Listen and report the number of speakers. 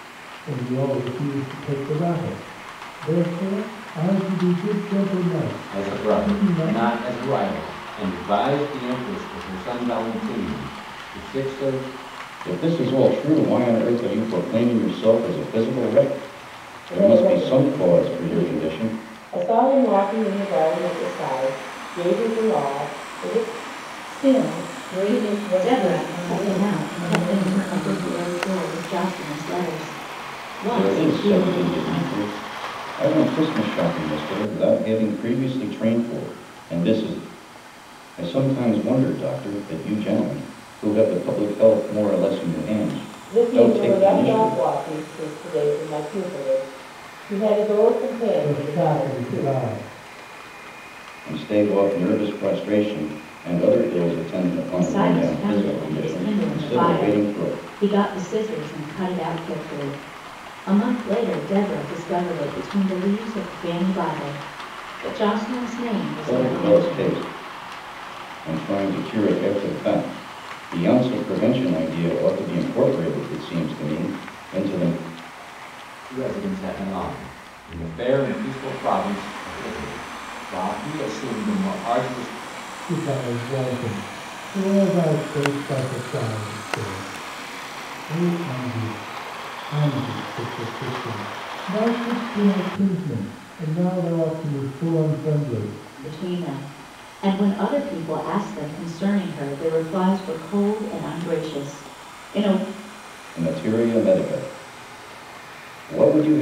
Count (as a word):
six